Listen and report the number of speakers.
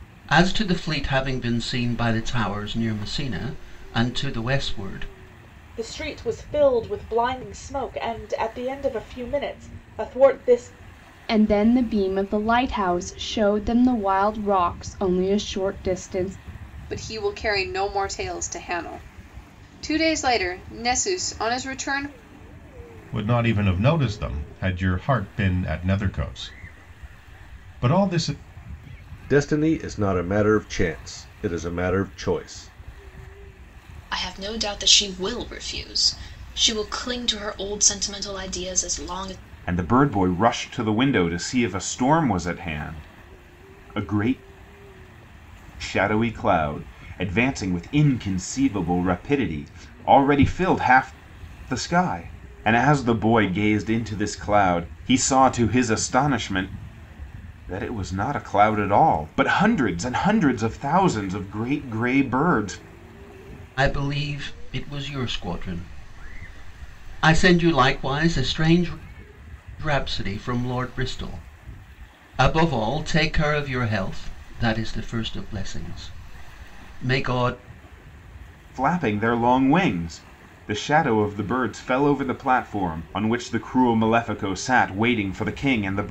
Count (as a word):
eight